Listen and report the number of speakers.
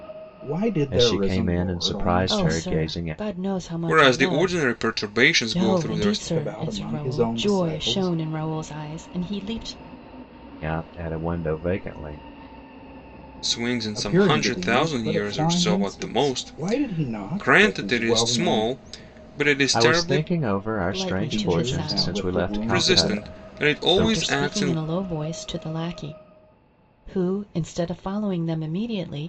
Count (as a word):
four